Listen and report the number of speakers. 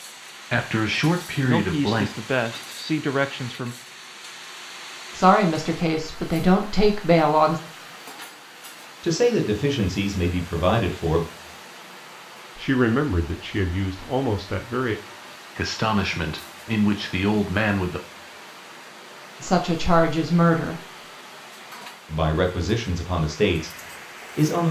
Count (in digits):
5